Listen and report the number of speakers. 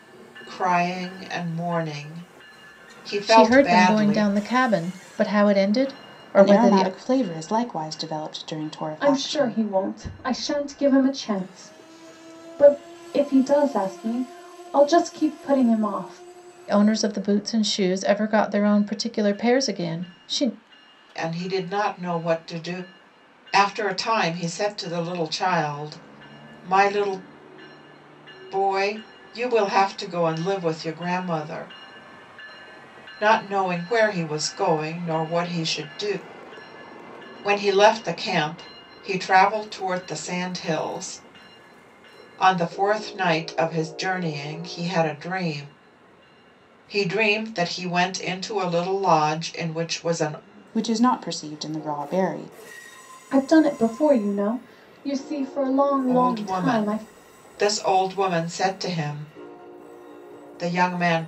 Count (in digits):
4